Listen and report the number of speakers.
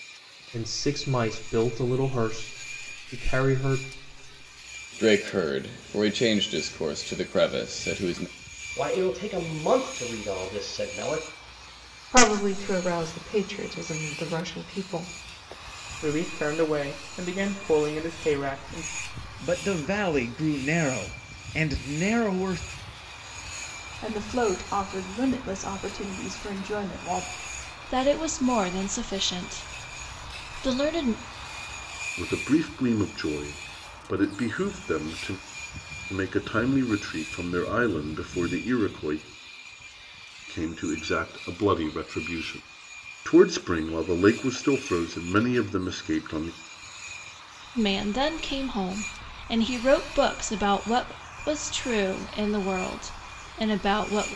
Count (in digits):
9